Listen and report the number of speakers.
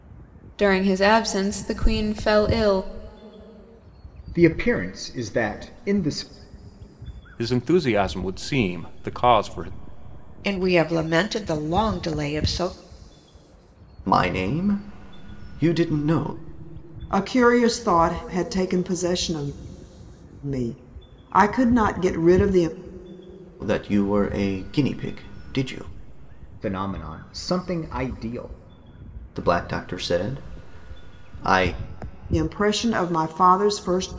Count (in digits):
6